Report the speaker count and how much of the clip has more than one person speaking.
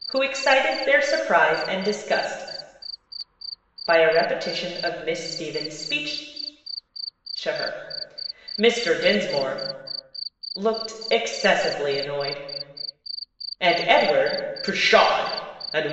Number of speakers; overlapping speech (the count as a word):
one, no overlap